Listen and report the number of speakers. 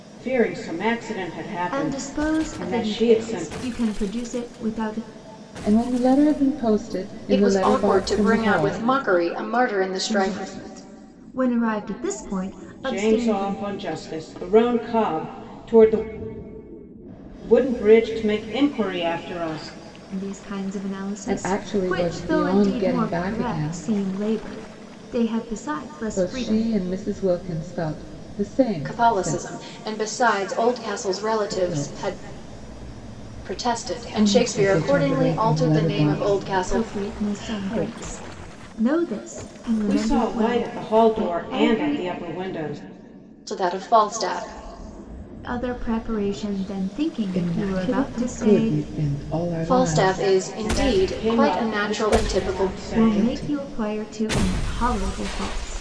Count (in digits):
4